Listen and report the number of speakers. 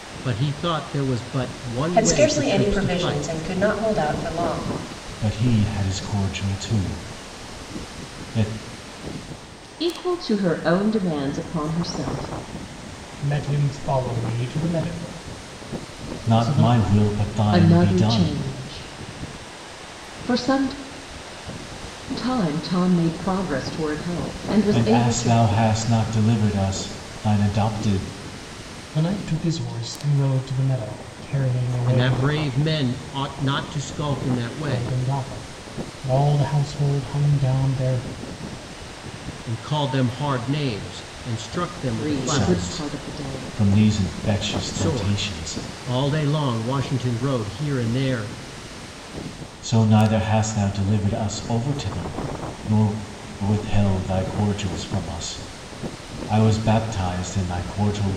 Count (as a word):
five